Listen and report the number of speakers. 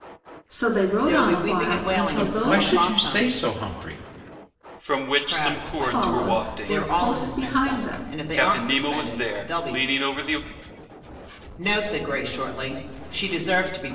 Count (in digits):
4